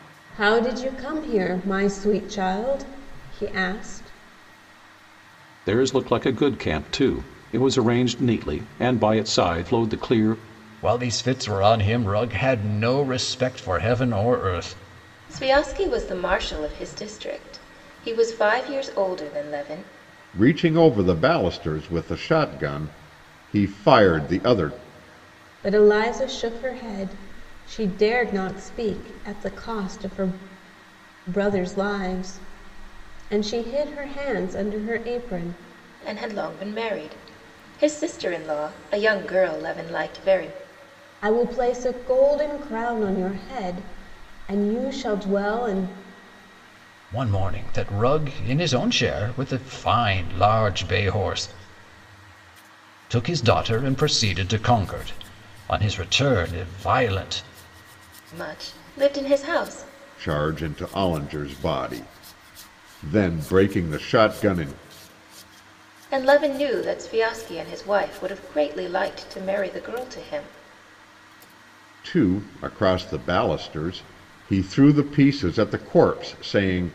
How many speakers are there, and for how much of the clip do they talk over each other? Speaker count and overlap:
5, no overlap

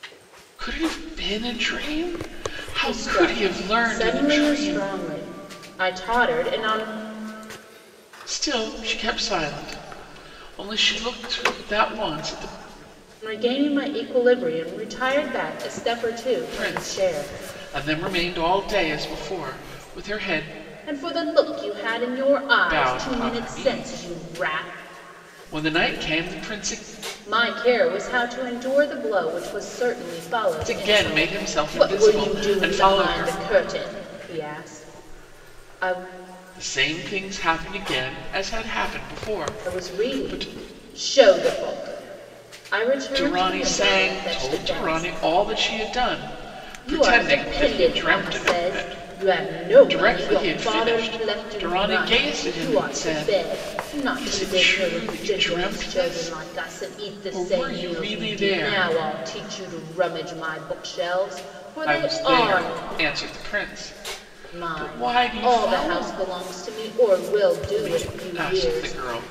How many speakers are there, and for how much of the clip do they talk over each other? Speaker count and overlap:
2, about 36%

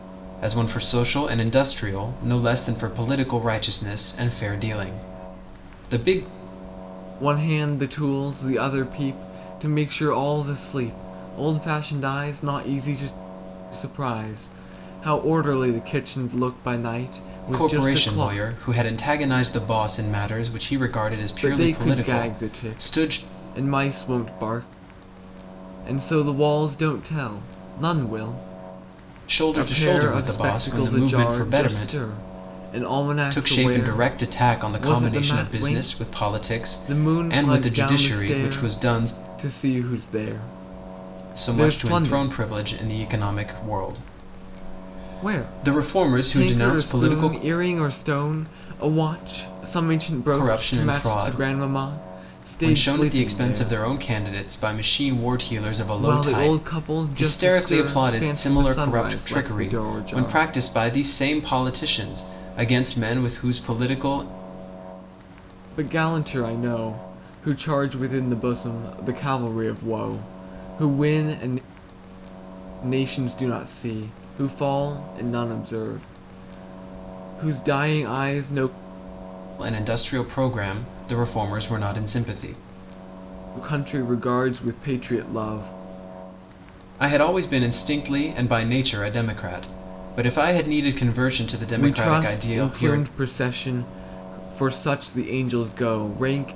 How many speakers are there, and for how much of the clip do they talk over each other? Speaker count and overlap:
2, about 23%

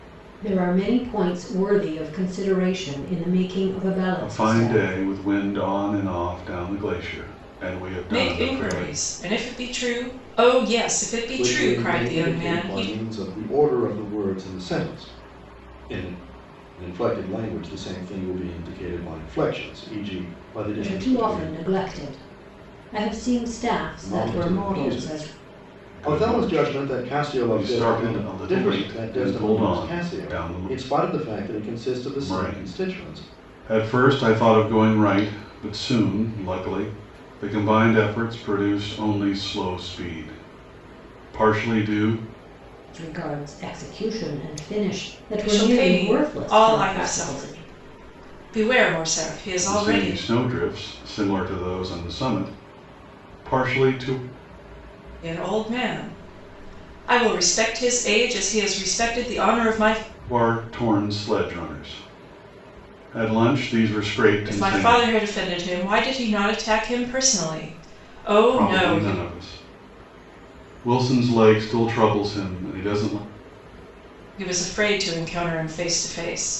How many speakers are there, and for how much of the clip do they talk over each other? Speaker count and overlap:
4, about 20%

